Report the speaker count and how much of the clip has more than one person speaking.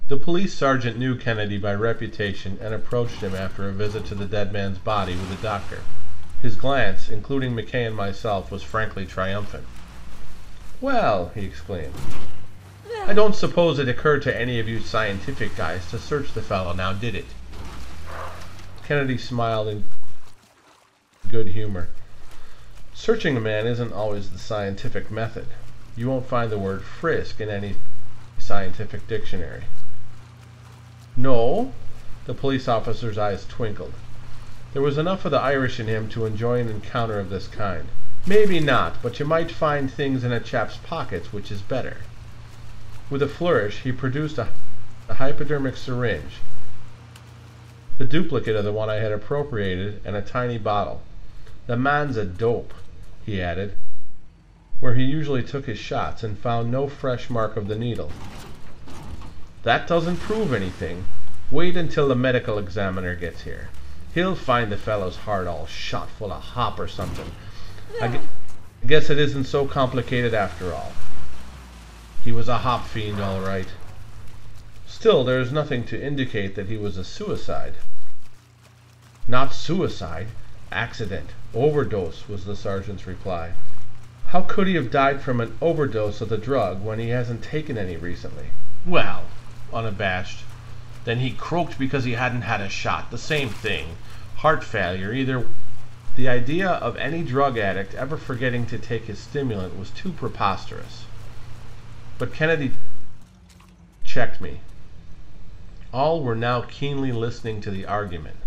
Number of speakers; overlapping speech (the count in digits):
1, no overlap